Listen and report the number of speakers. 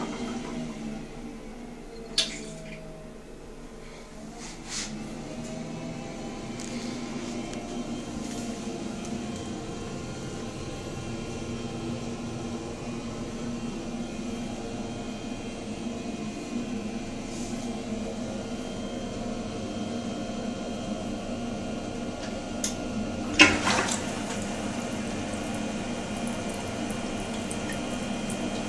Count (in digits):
0